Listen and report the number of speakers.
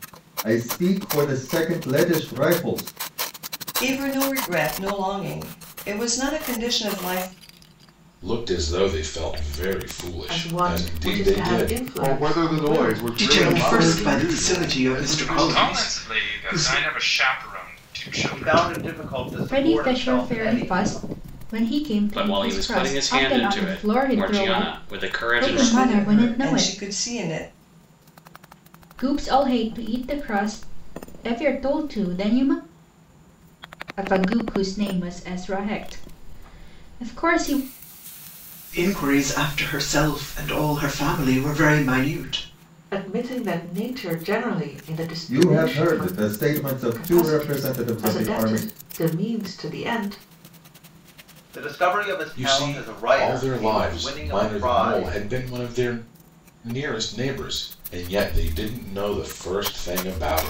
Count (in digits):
10